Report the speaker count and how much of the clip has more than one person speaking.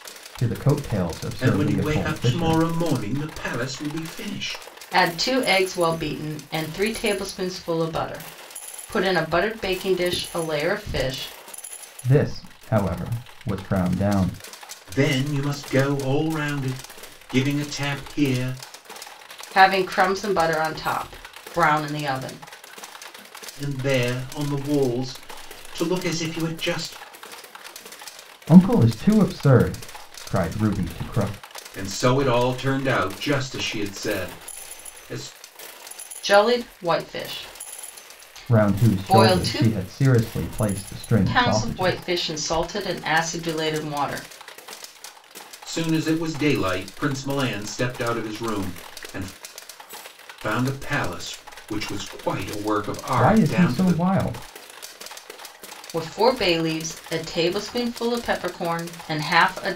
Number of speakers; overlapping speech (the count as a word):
three, about 7%